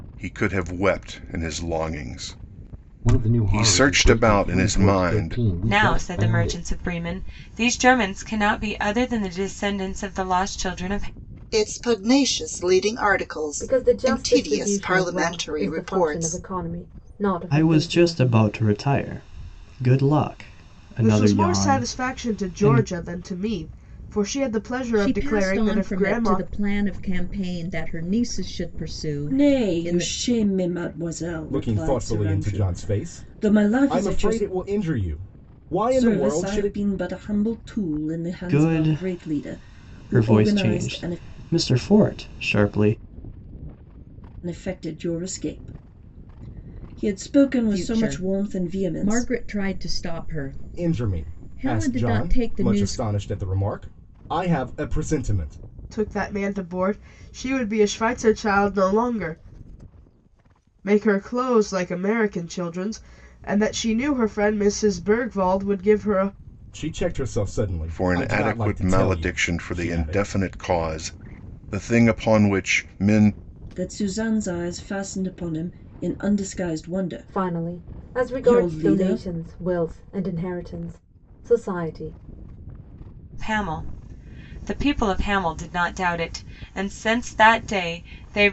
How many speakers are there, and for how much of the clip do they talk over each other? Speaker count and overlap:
ten, about 30%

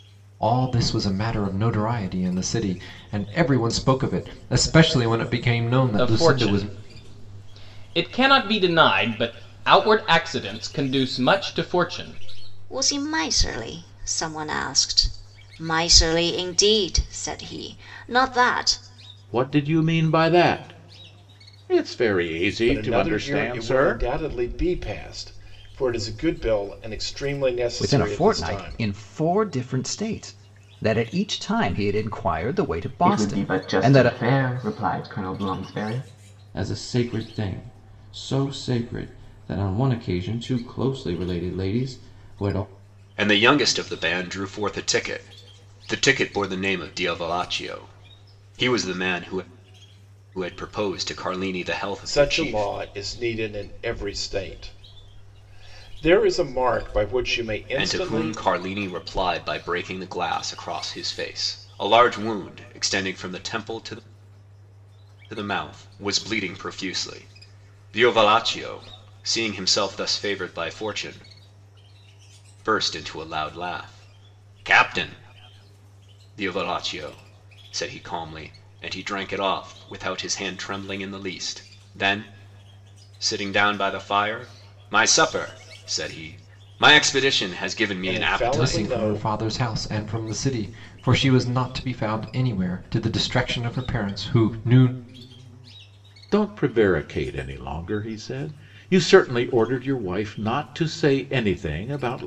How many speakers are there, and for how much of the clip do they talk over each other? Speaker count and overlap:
nine, about 7%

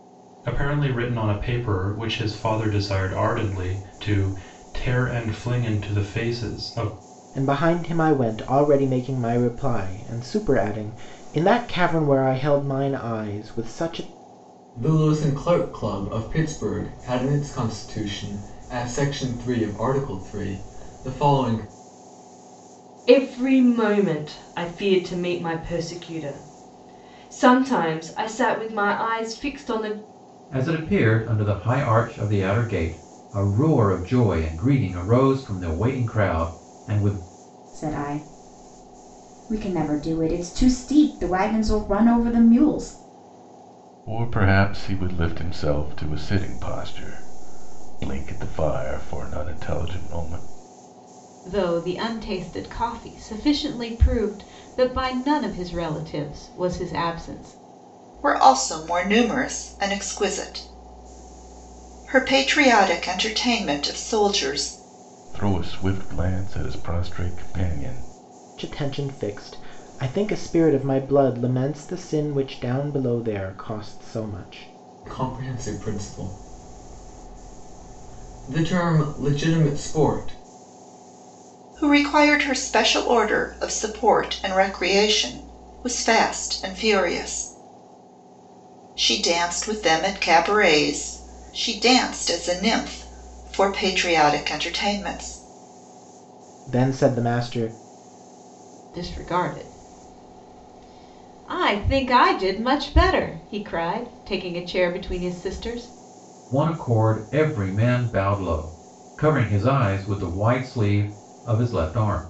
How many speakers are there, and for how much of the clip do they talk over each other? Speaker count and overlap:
nine, no overlap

